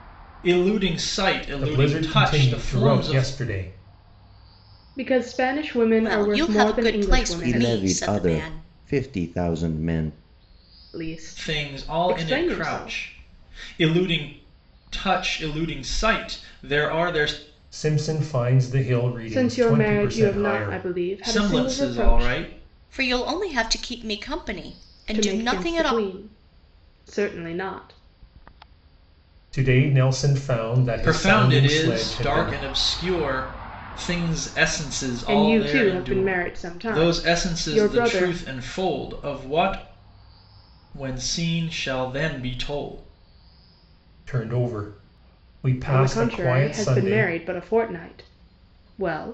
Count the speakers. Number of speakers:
five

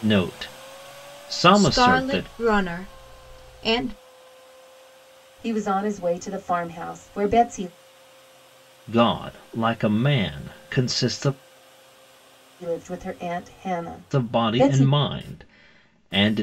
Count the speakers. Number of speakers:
three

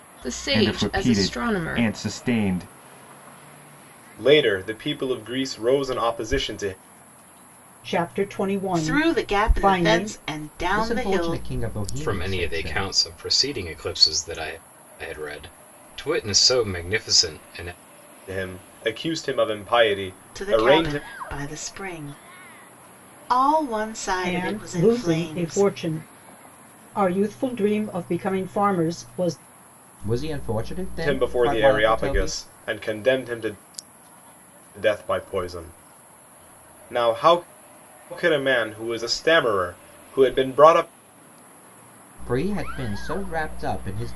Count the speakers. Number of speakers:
seven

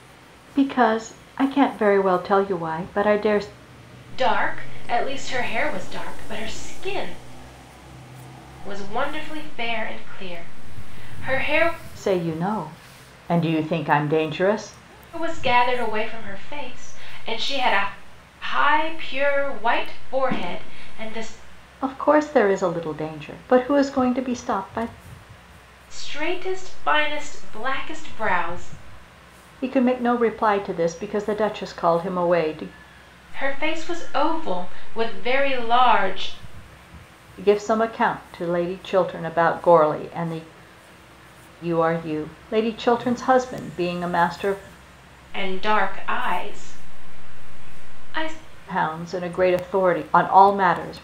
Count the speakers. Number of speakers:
two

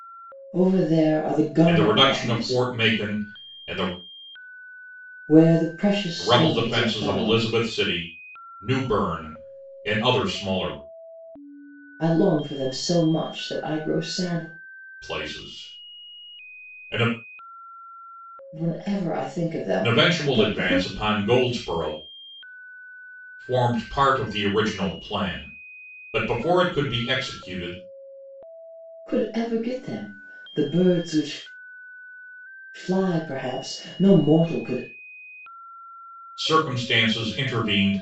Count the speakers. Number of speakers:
two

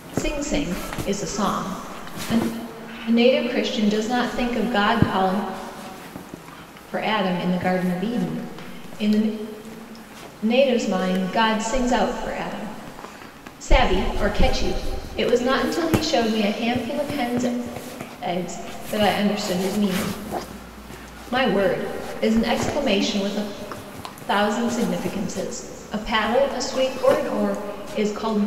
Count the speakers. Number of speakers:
one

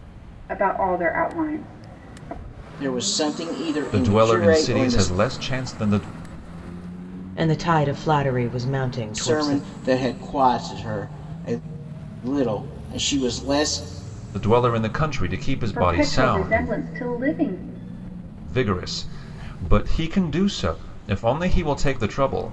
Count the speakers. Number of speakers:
four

